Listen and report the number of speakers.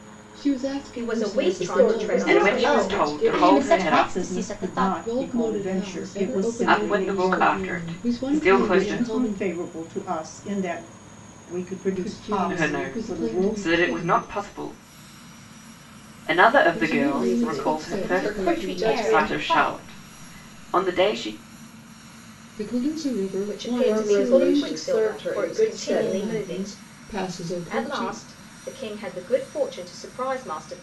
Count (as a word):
six